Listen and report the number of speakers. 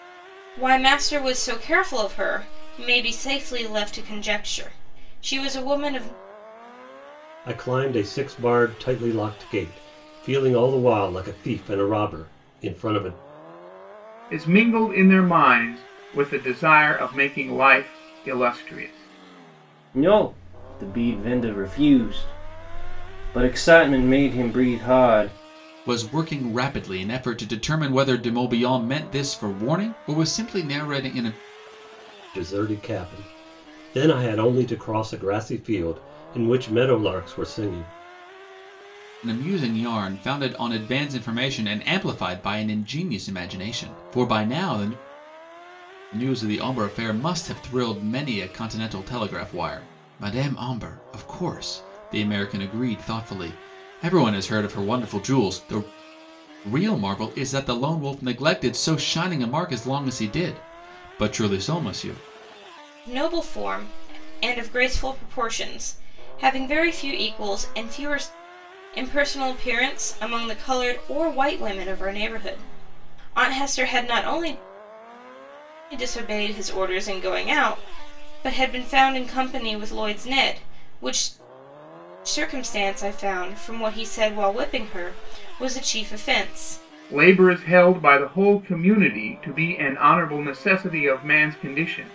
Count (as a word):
five